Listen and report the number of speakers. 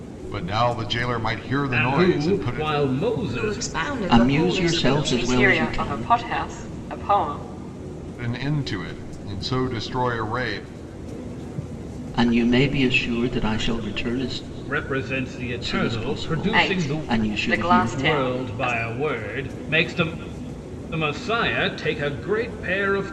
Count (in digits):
5